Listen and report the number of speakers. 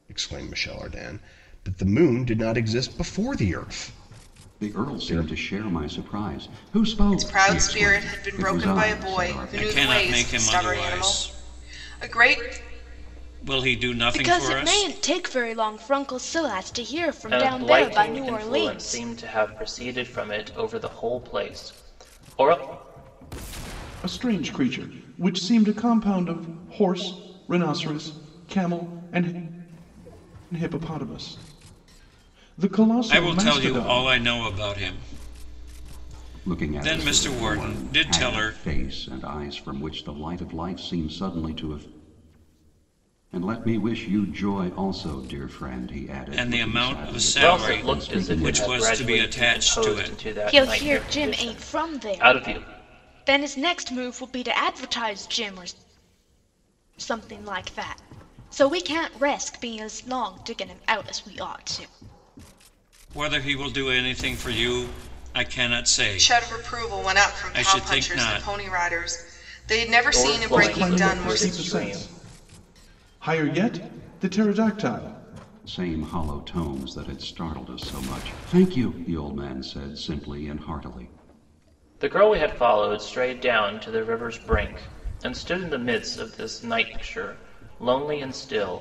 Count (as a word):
seven